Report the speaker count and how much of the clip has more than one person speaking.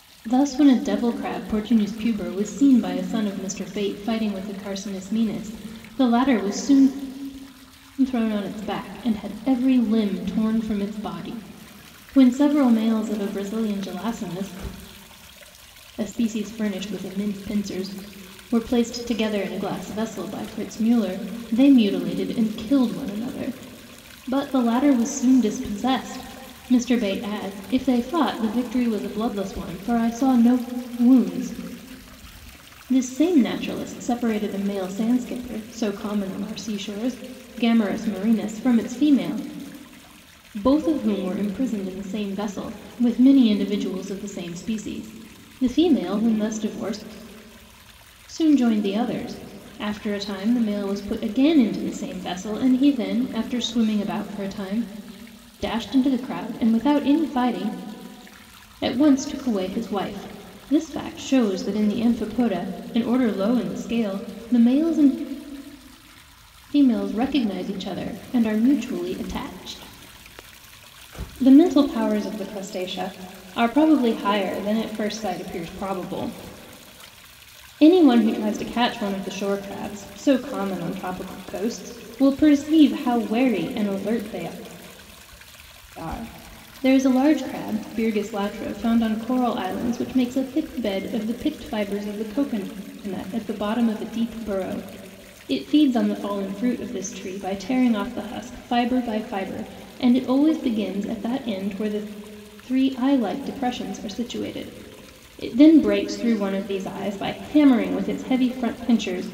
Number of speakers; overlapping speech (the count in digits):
1, no overlap